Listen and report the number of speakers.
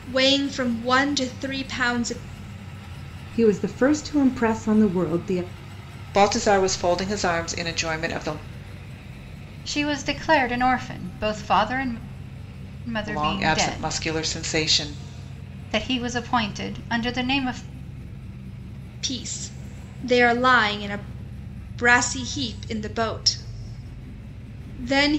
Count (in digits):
4